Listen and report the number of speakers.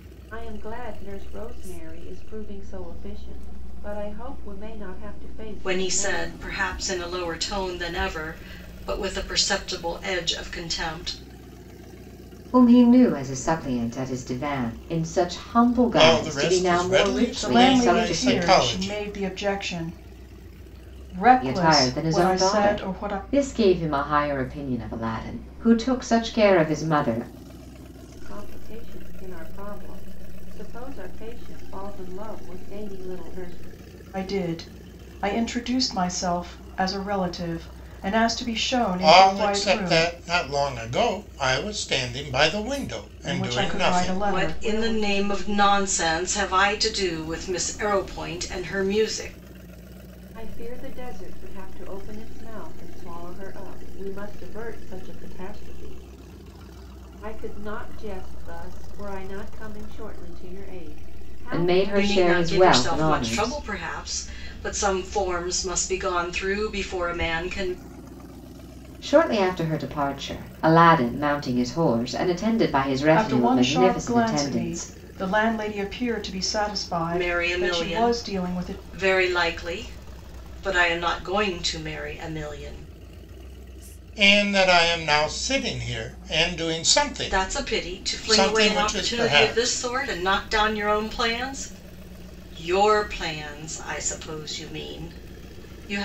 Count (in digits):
5